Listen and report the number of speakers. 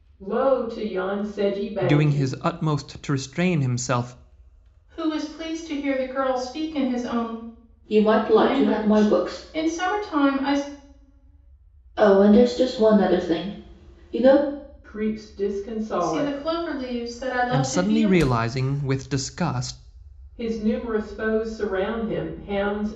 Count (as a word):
four